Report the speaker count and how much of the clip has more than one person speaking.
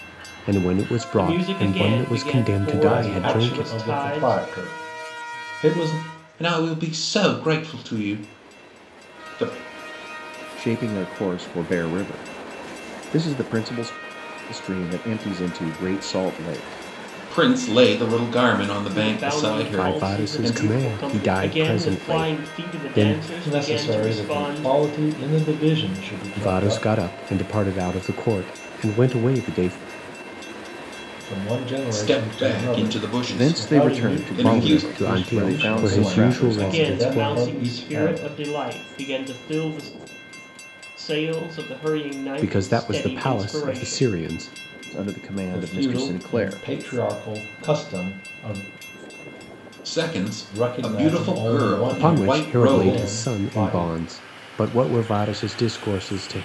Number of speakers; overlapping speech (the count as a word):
five, about 40%